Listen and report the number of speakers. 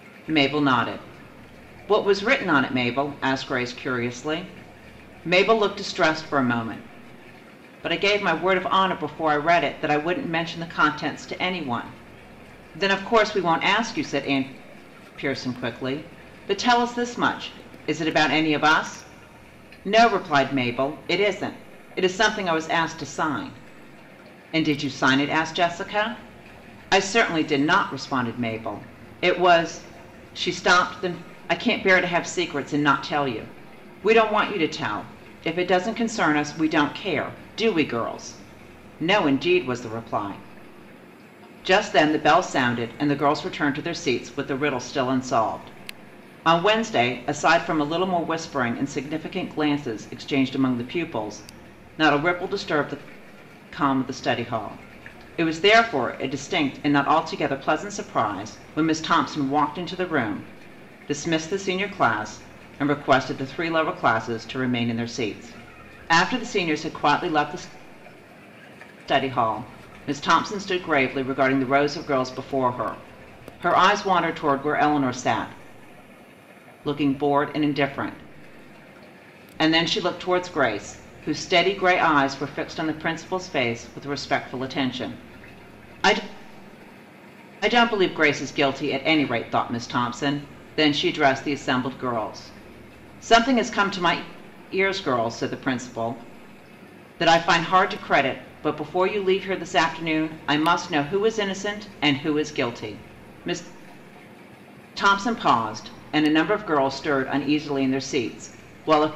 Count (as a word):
one